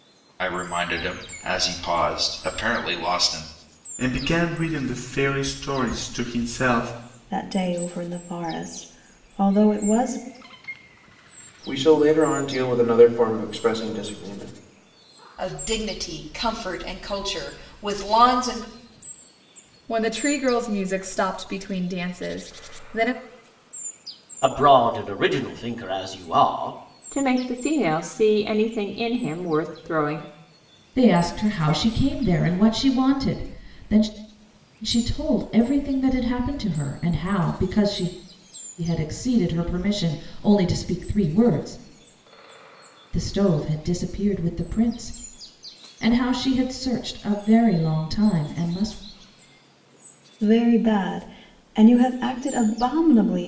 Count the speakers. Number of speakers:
9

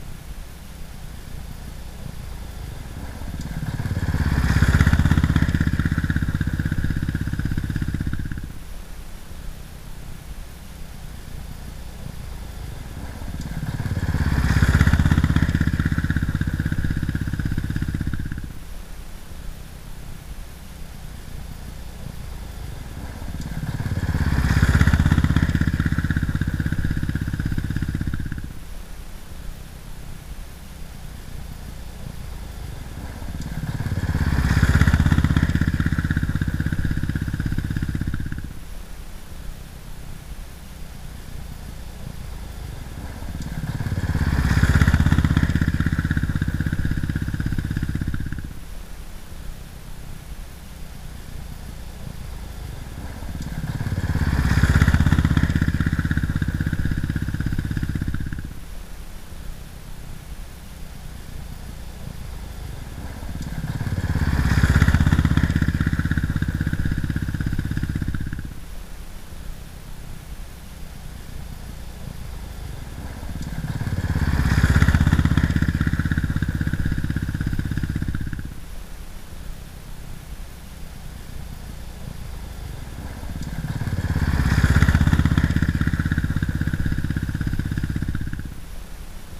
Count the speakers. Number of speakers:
0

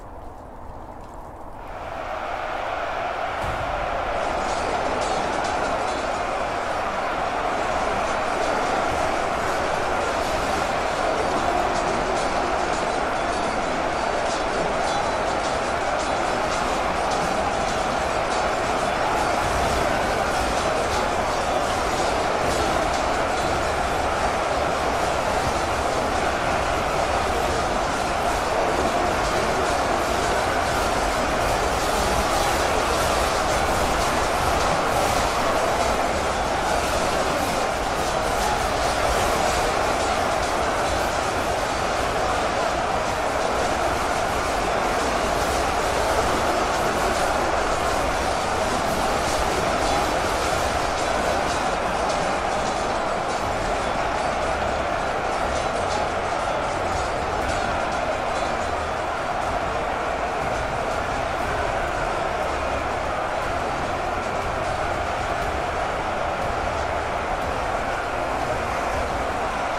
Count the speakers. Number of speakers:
0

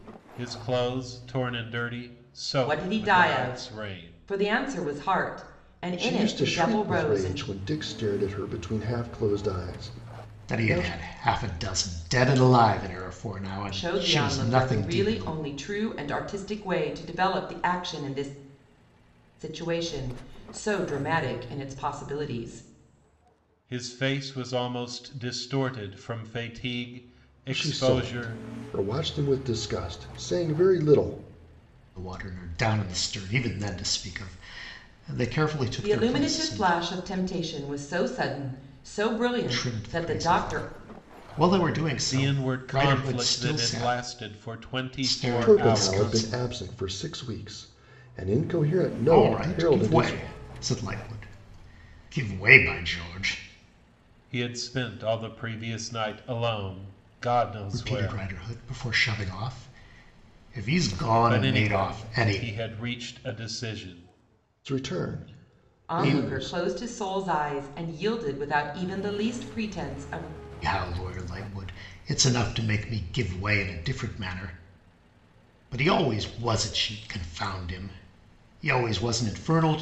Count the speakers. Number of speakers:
4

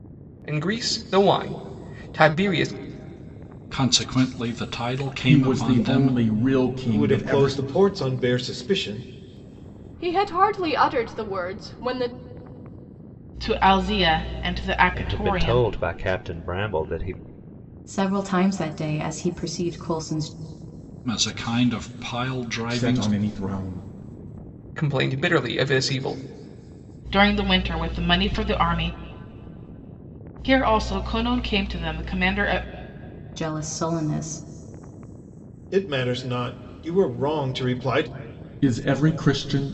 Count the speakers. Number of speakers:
8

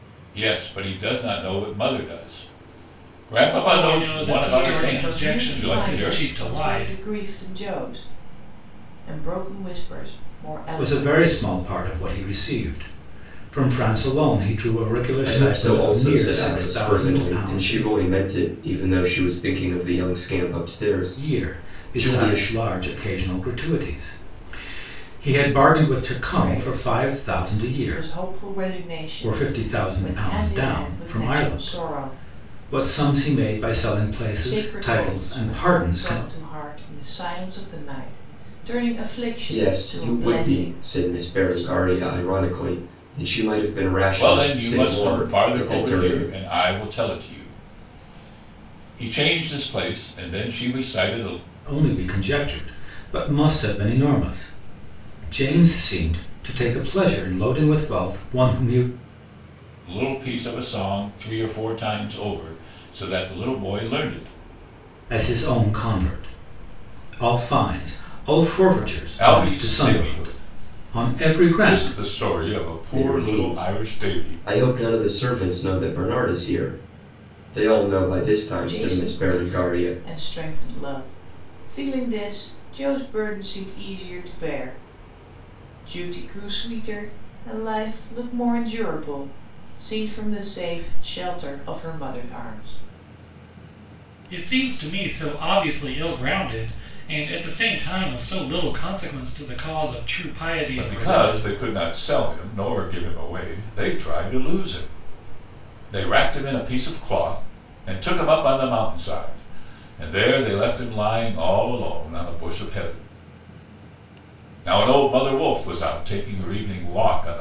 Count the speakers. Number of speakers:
5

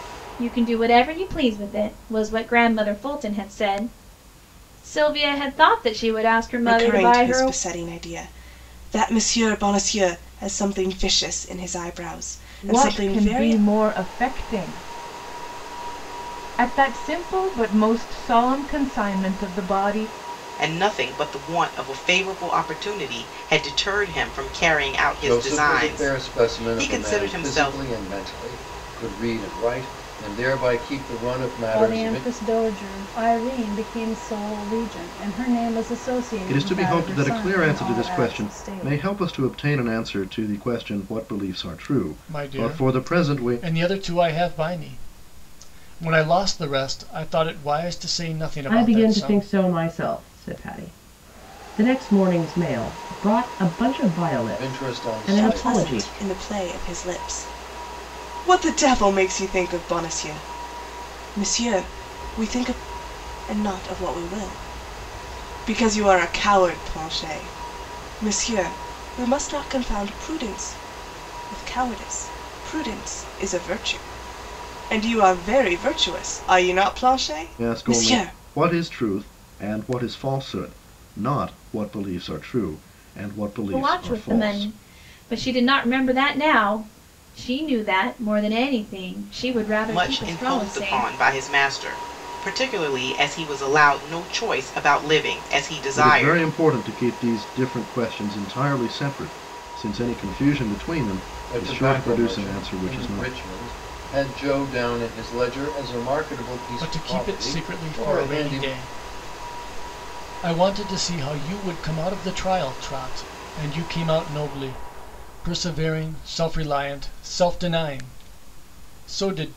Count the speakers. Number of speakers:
9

